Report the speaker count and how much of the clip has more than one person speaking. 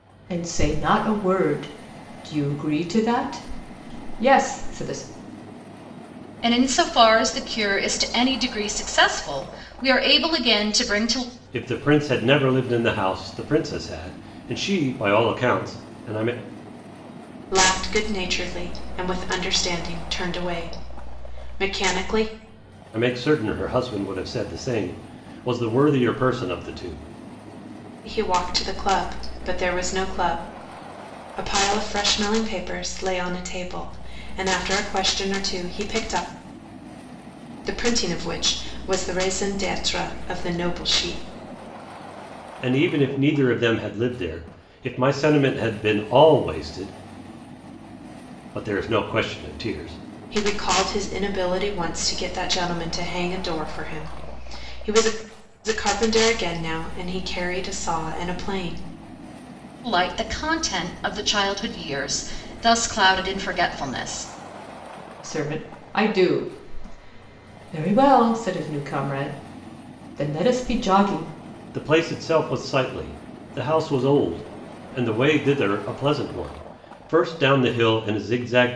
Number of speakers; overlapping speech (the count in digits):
4, no overlap